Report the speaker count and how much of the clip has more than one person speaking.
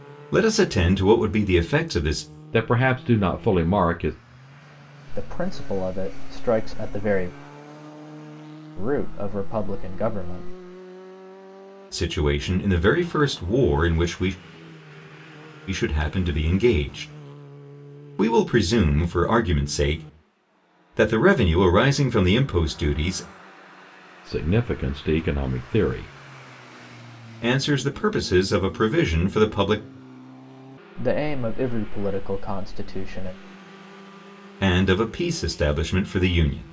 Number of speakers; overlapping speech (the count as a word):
three, no overlap